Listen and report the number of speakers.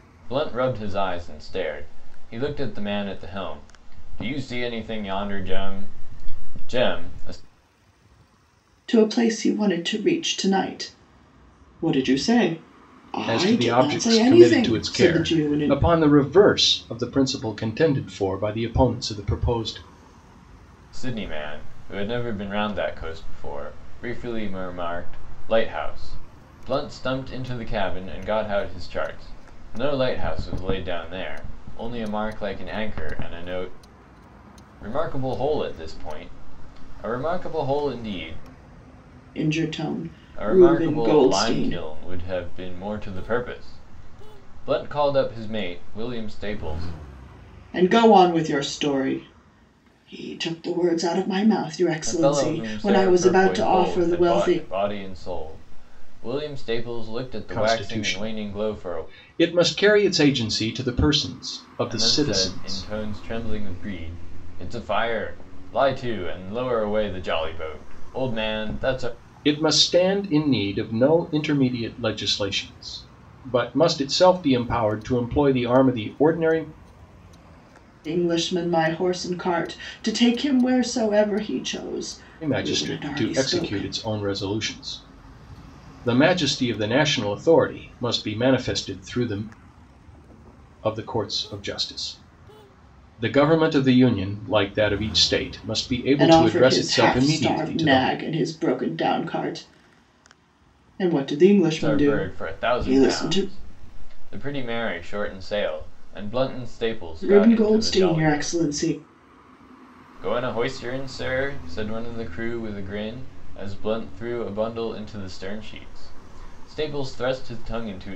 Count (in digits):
3